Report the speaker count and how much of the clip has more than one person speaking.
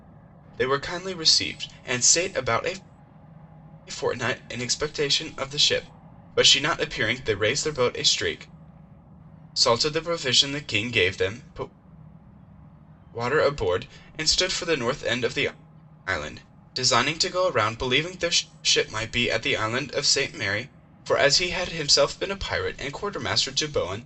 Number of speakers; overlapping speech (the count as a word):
one, no overlap